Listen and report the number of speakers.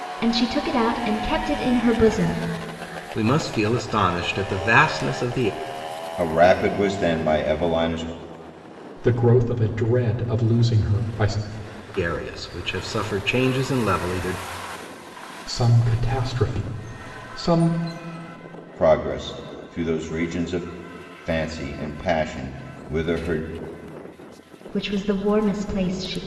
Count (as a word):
four